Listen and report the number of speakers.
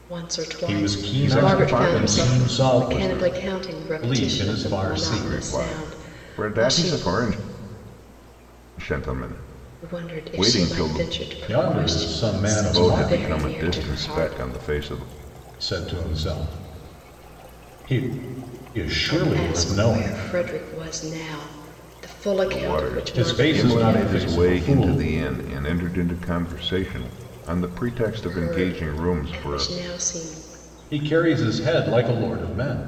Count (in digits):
3